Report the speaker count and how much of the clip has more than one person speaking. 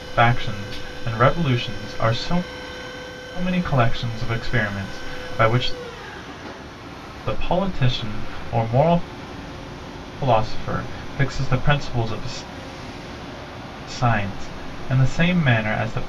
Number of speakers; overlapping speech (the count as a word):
one, no overlap